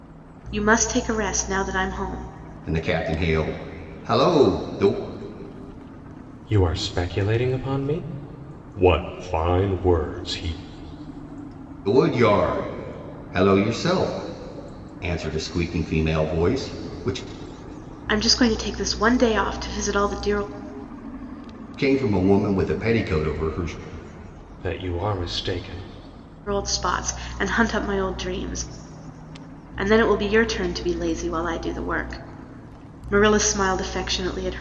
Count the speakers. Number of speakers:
three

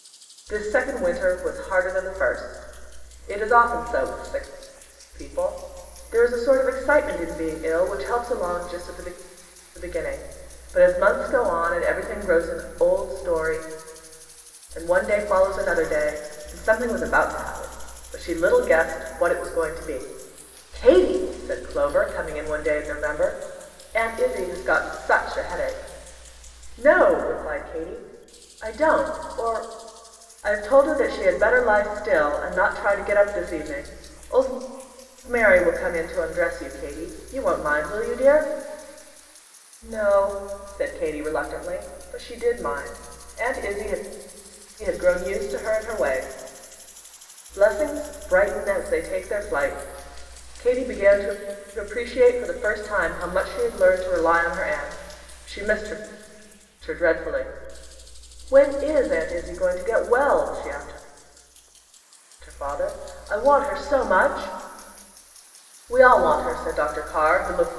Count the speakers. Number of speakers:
one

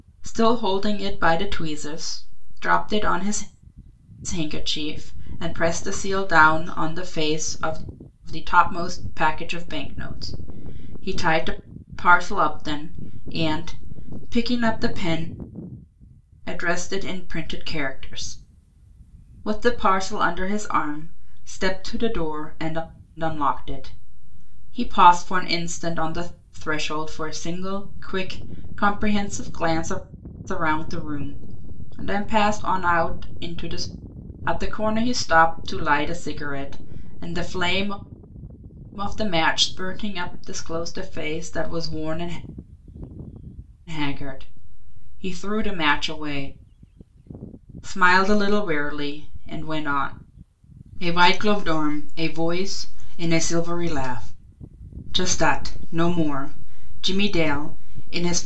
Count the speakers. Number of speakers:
one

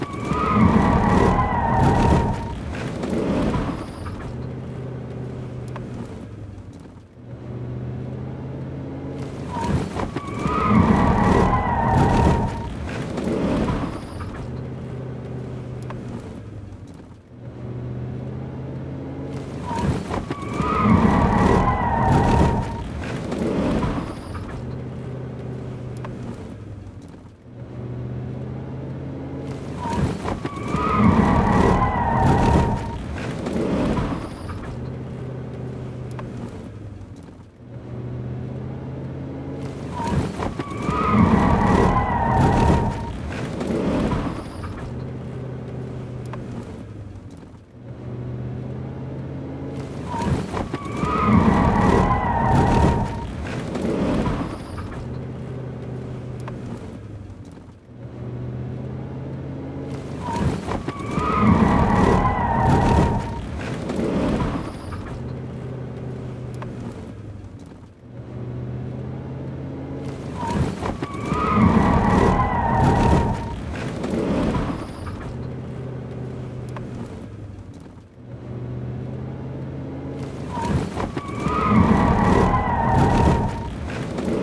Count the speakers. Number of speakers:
zero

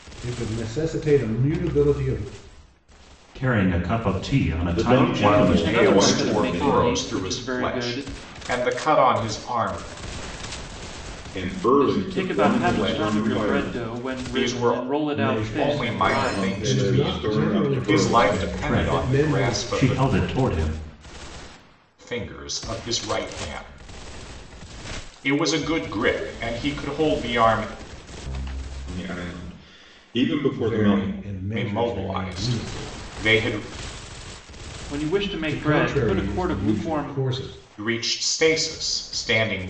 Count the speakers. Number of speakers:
five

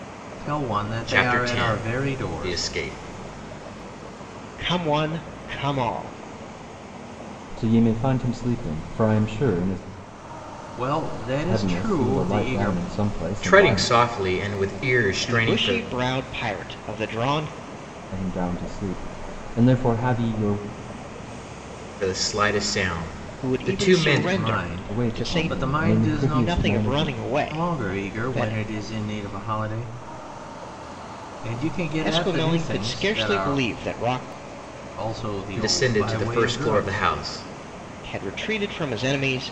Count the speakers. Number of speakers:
four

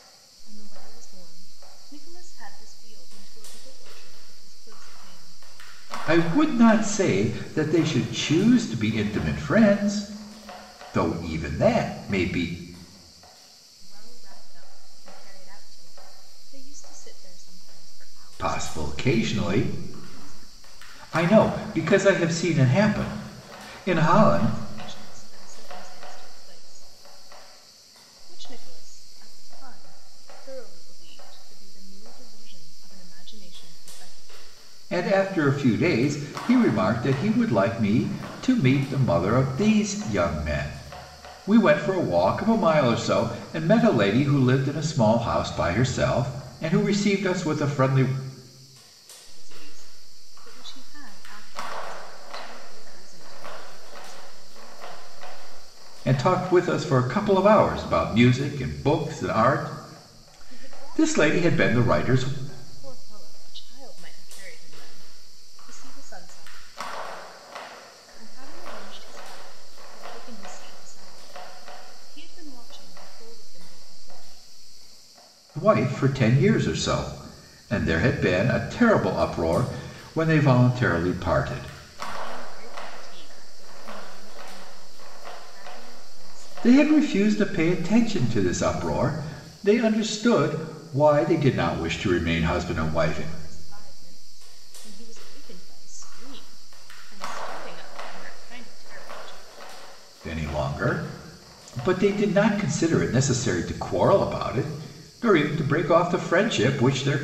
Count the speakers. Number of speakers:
two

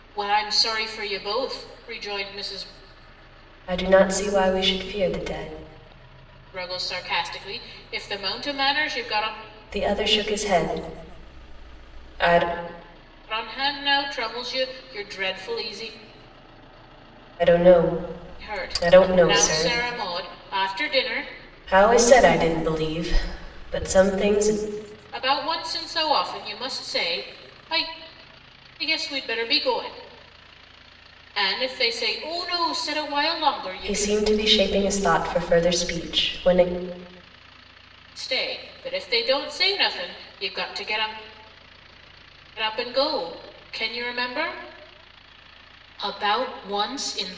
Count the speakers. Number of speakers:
two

